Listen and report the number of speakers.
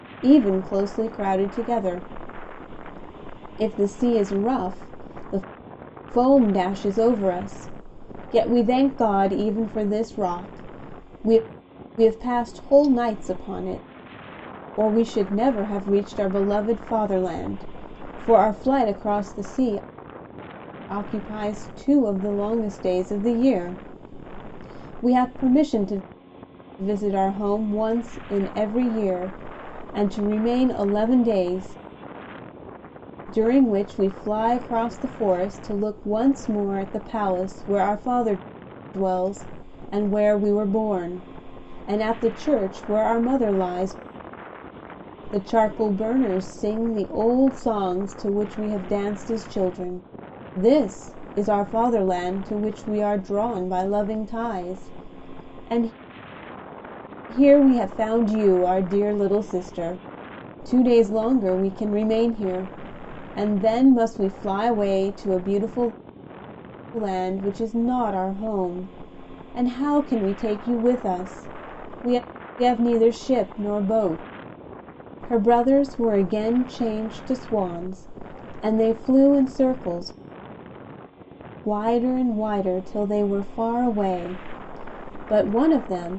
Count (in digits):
1